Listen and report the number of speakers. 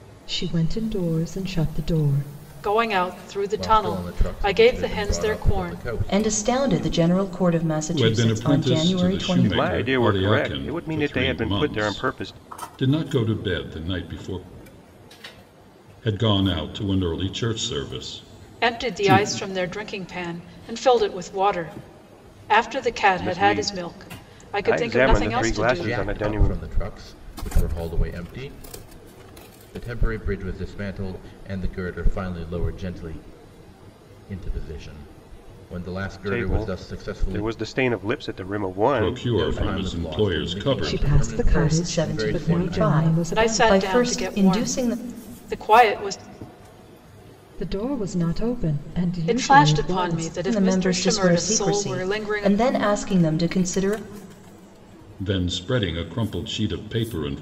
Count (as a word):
six